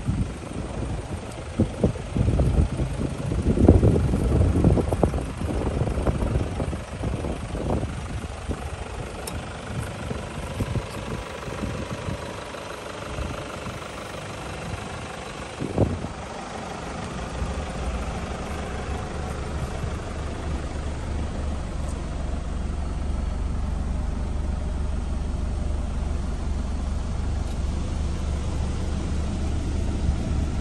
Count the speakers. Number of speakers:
0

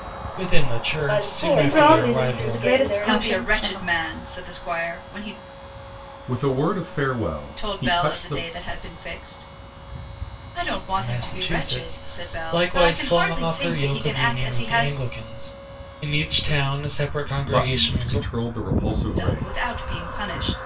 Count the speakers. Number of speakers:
5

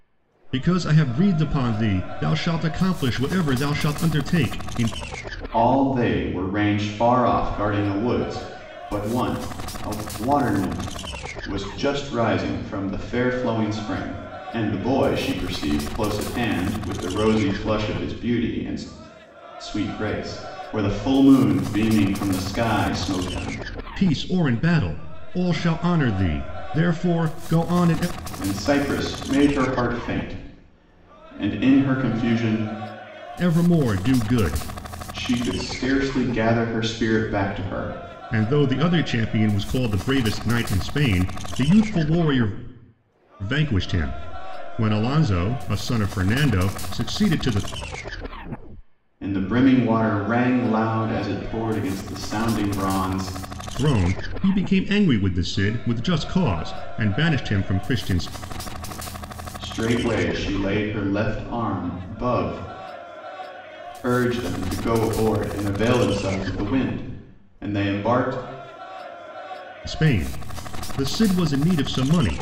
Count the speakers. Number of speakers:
2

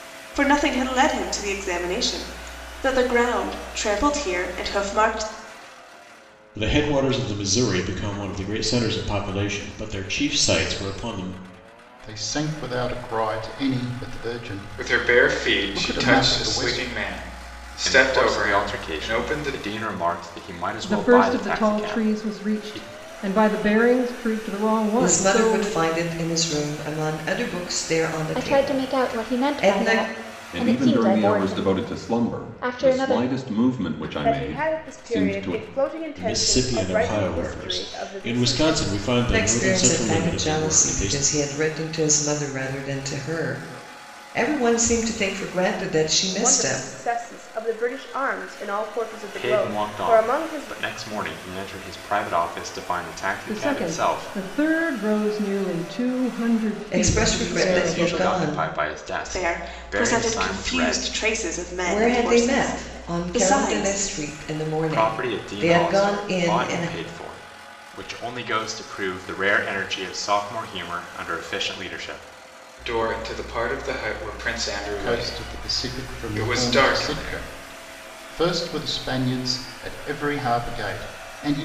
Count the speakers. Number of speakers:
10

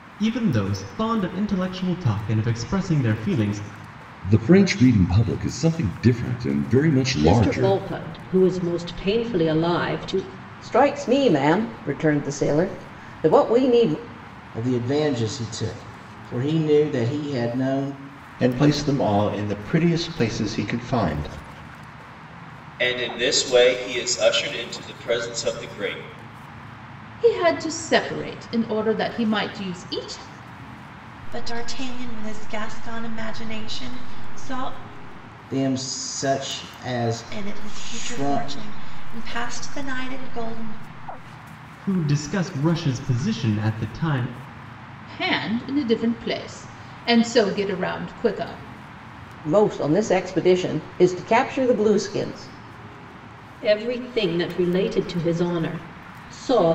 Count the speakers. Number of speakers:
9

